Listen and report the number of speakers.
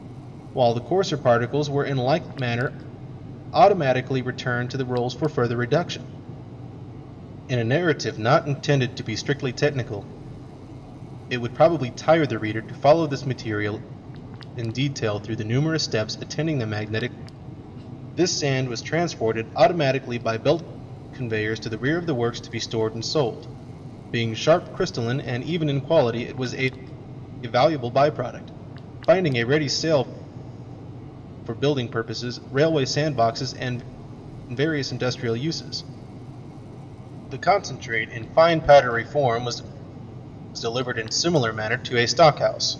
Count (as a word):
one